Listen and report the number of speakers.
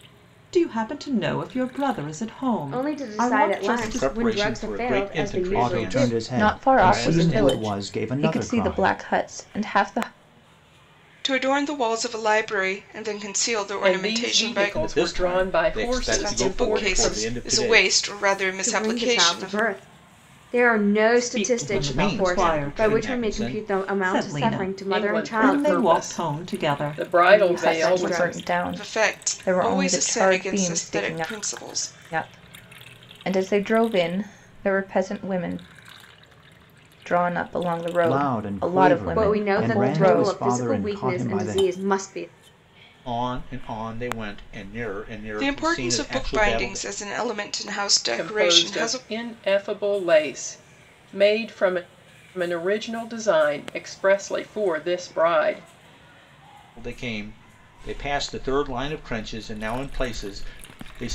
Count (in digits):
7